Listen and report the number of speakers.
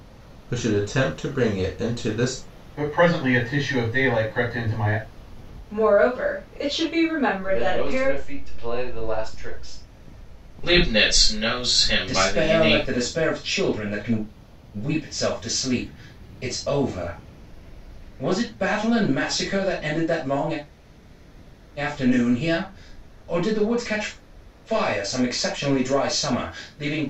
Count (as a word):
six